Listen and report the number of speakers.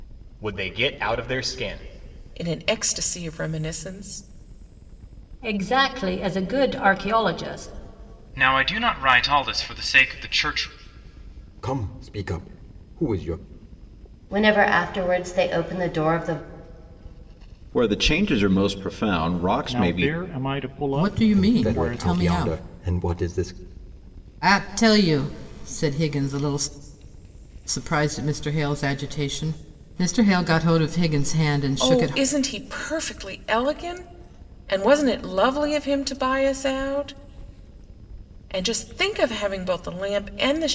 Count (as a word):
nine